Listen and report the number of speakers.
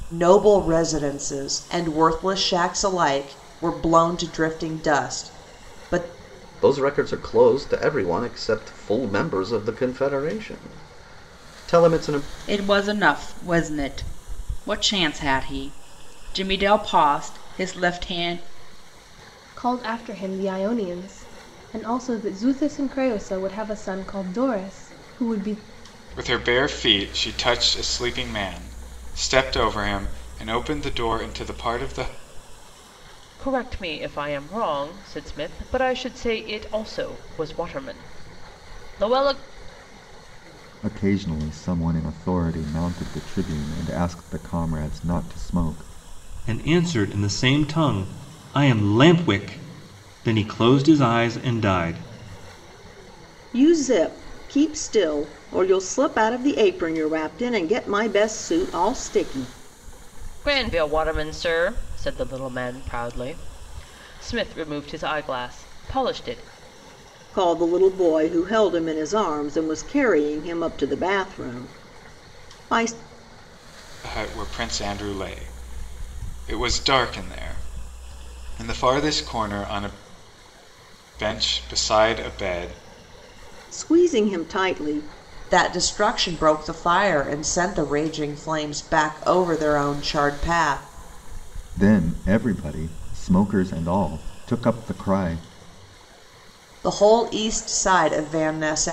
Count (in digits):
9